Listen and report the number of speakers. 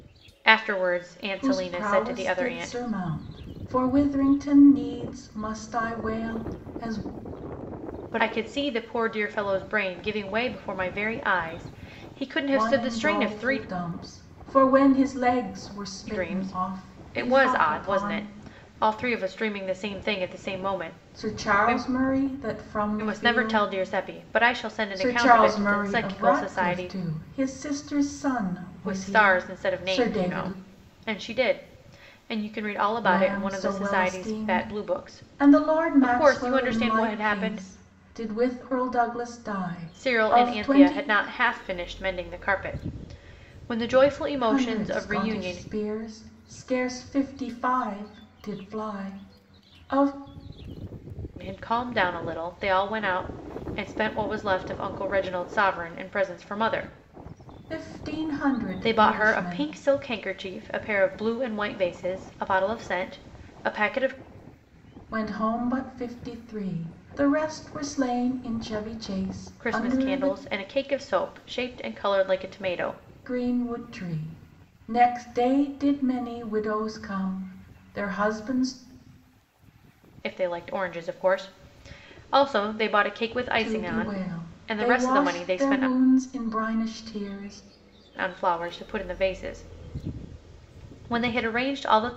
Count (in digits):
2